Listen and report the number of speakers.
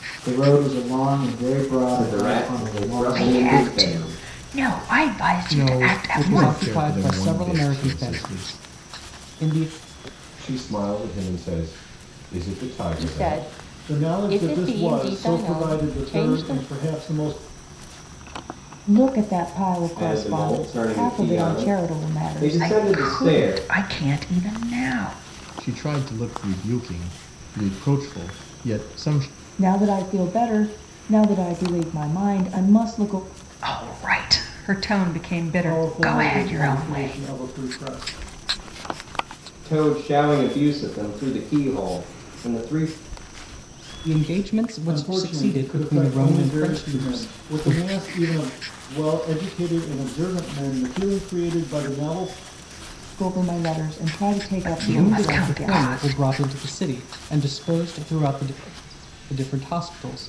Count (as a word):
nine